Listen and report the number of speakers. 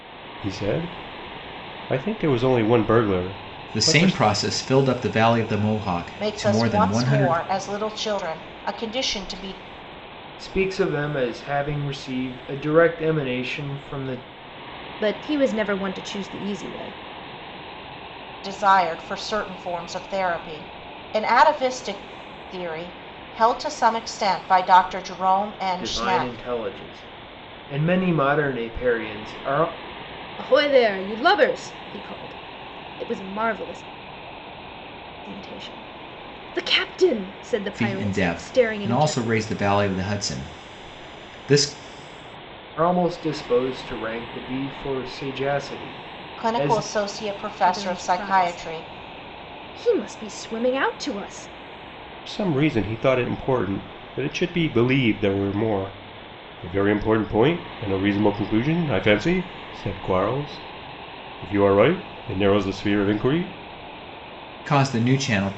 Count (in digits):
5